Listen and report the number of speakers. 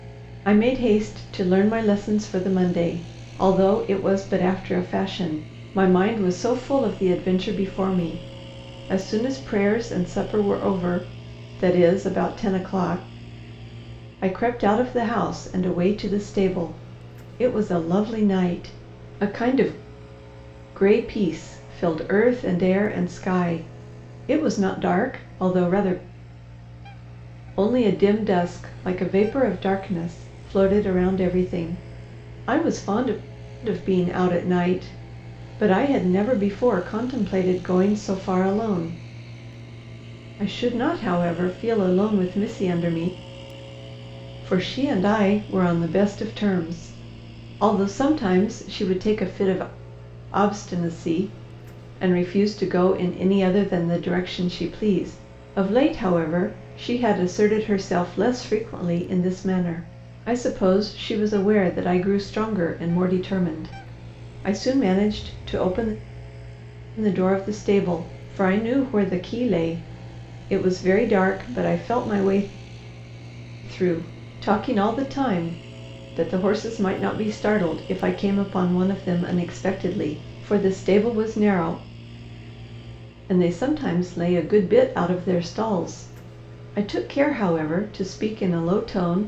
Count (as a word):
one